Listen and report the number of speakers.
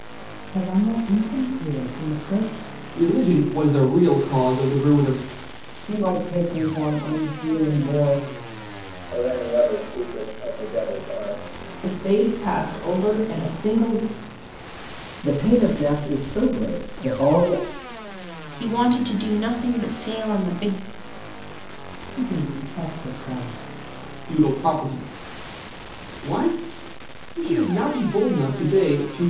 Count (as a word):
seven